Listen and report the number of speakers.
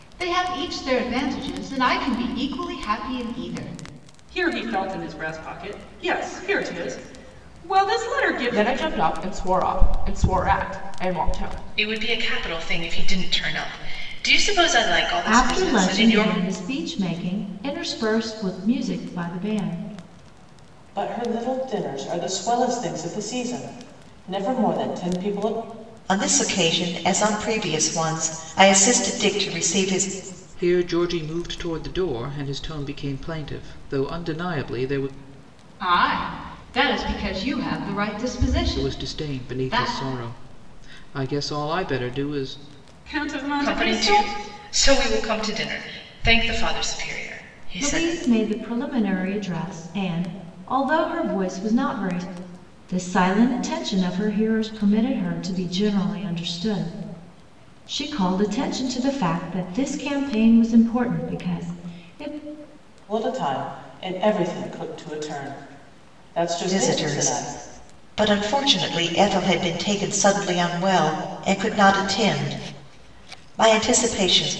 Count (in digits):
8